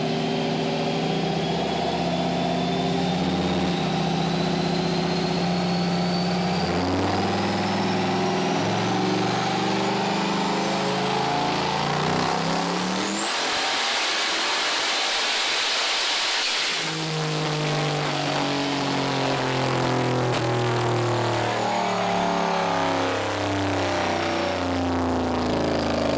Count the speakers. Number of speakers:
zero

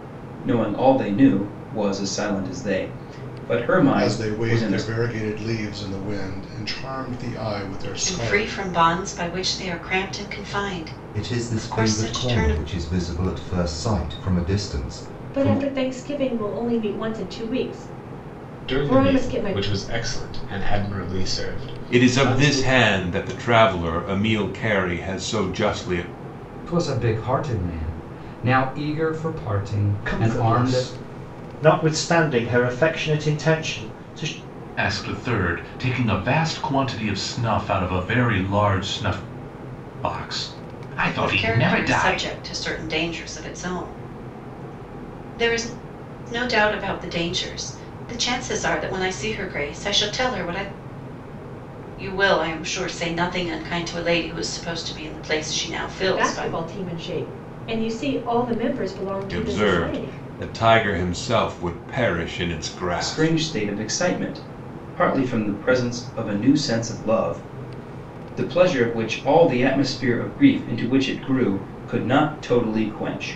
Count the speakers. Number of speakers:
ten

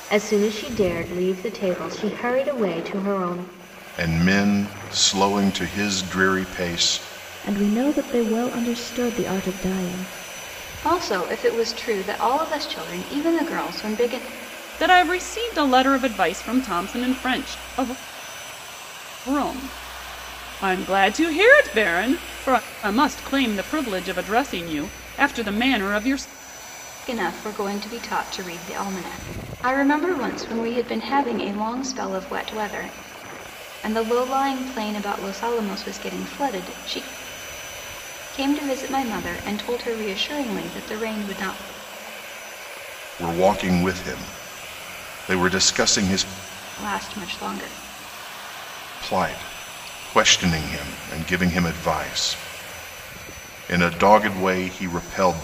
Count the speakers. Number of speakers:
five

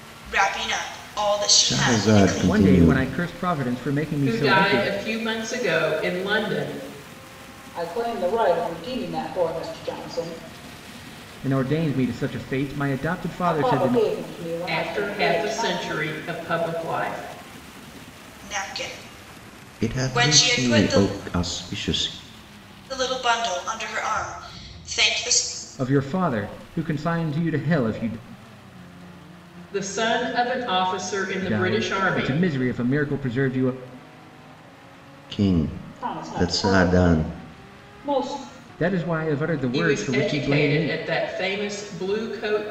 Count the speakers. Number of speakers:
five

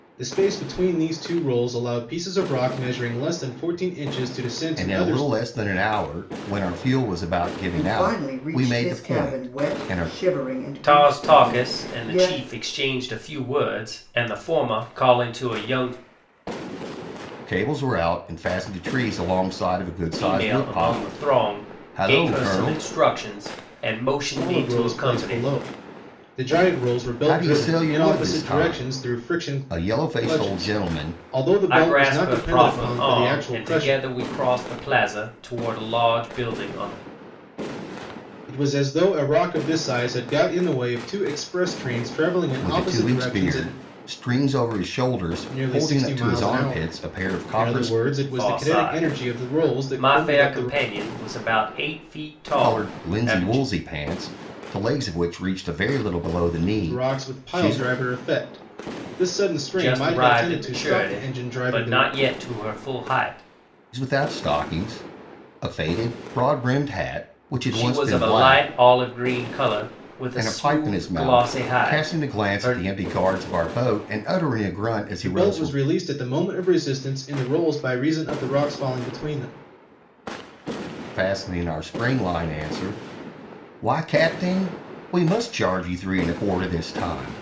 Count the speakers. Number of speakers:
four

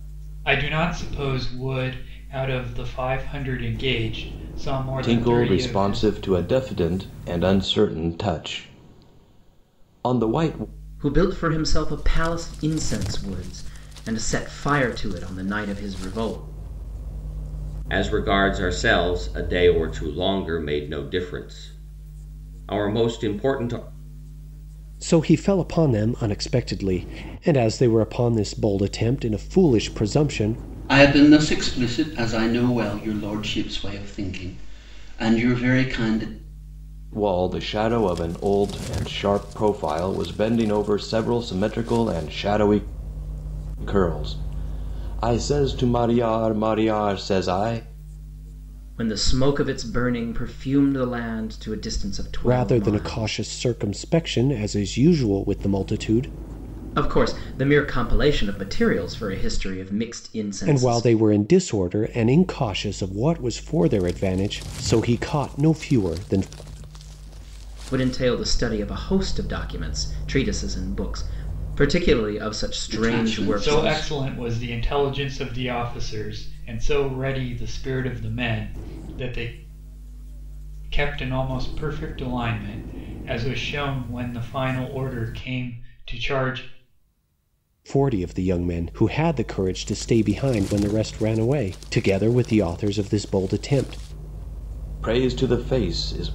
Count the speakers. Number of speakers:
six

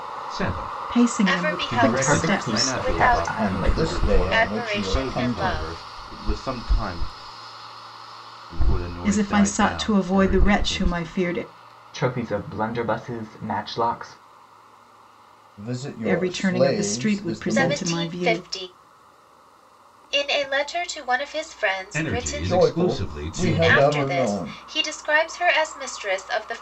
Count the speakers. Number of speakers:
six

